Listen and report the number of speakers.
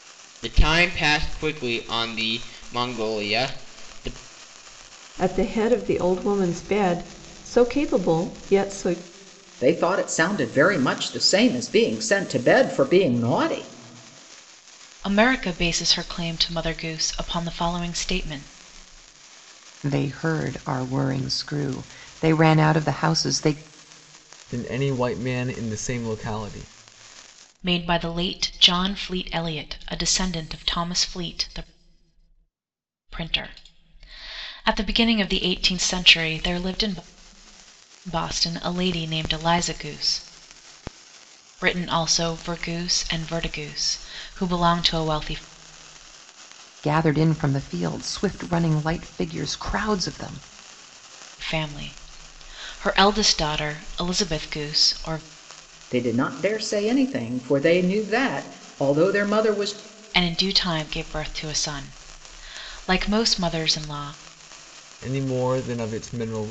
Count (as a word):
six